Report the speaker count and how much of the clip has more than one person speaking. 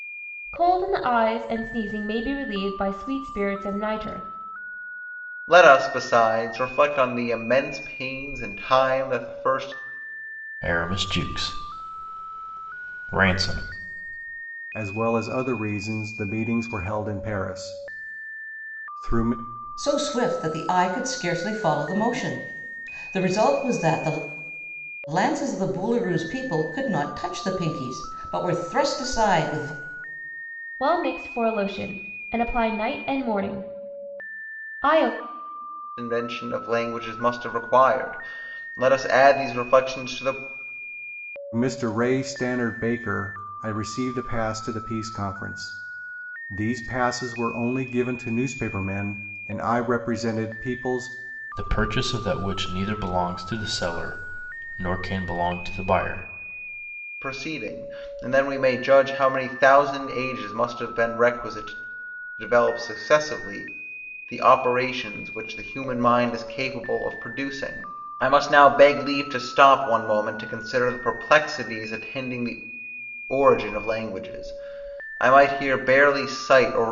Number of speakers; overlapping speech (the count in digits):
5, no overlap